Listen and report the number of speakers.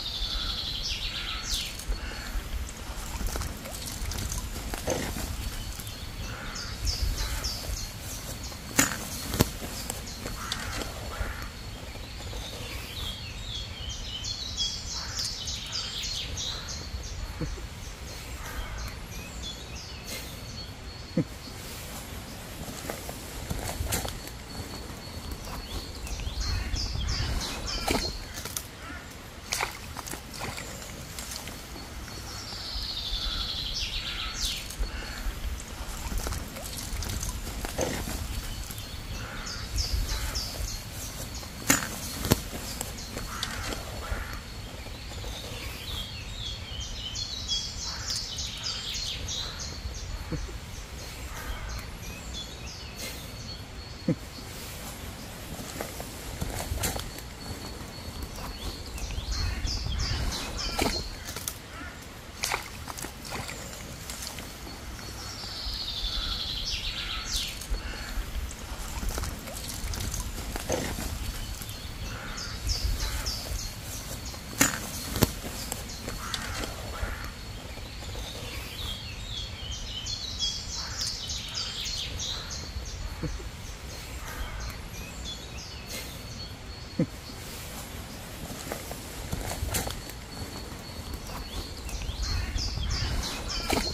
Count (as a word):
zero